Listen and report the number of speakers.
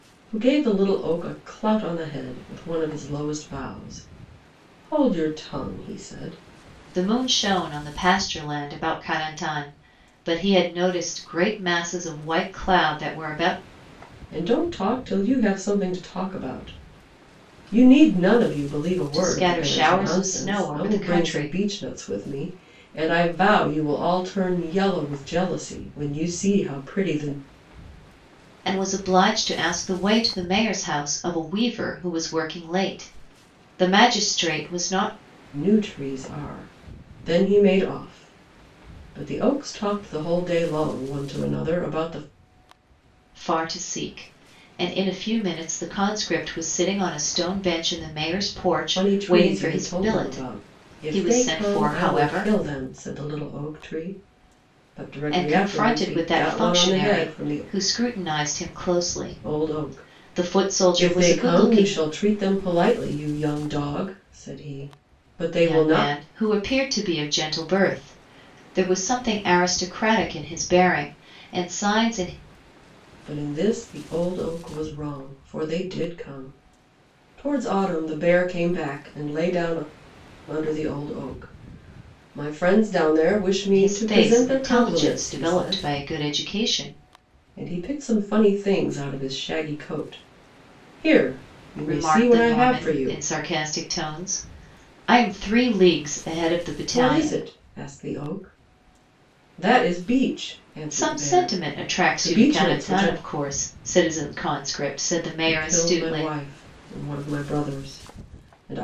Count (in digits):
2